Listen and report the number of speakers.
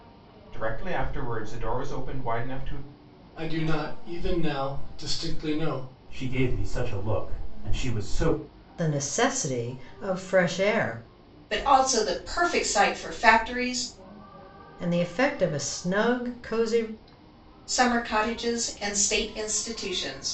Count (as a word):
five